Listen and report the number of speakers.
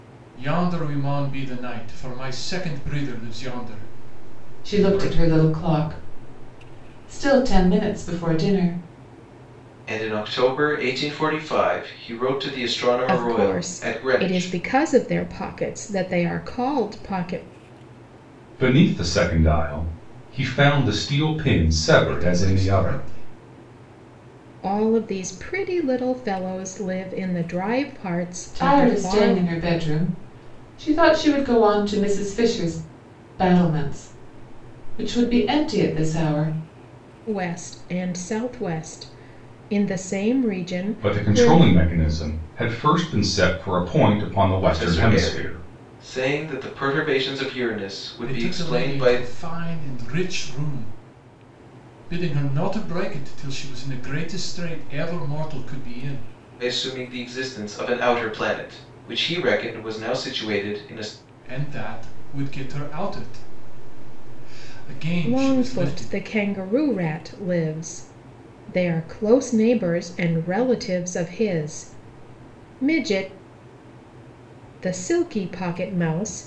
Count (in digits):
5